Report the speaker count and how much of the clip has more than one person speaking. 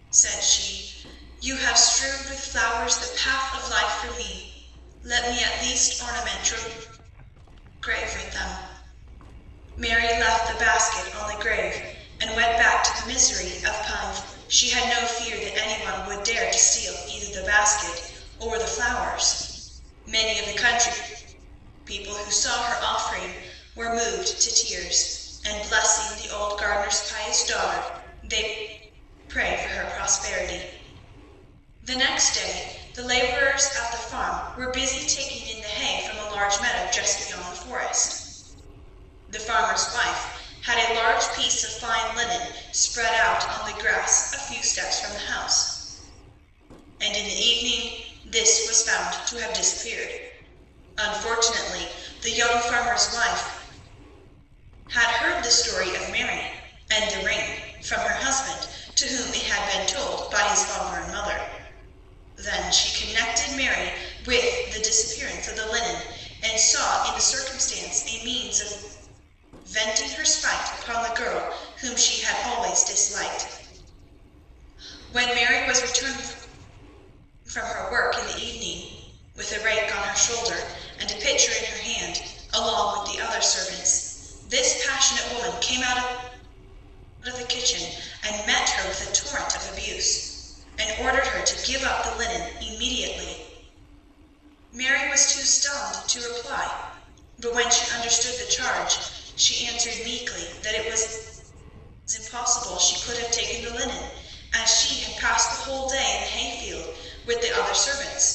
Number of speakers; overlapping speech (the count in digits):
1, no overlap